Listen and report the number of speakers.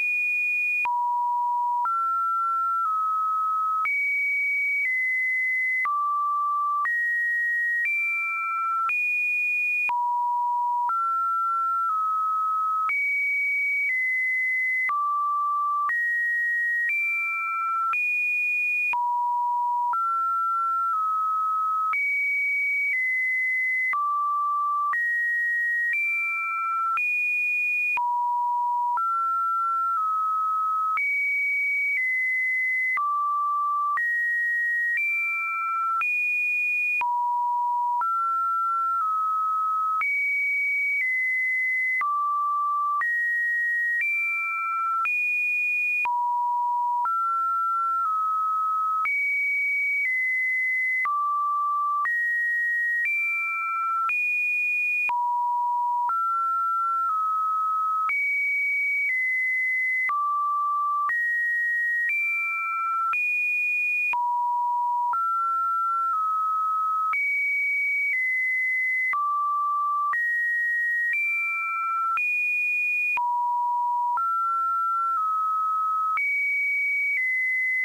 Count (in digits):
0